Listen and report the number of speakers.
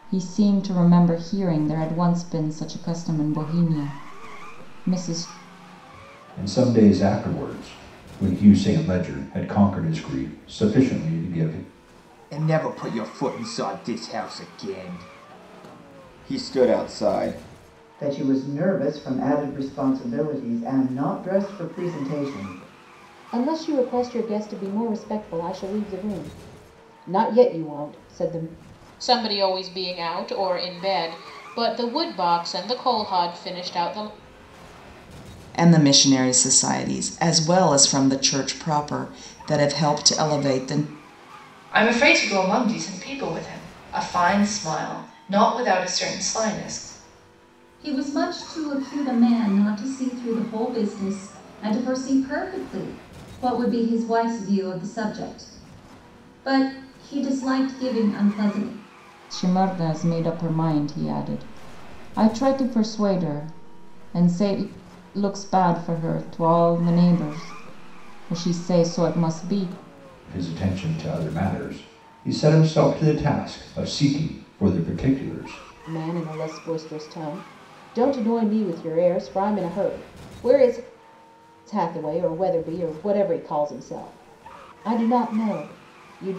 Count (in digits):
9